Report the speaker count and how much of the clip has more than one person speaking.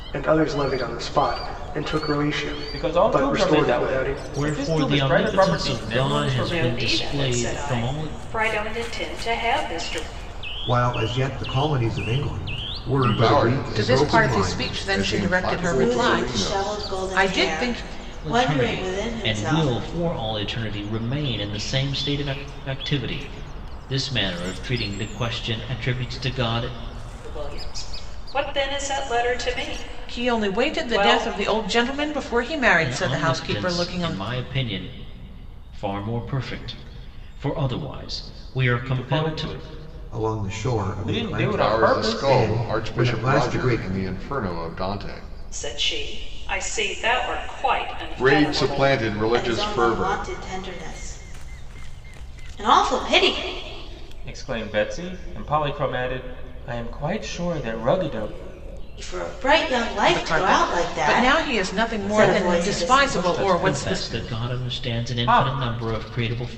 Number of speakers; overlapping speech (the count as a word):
eight, about 39%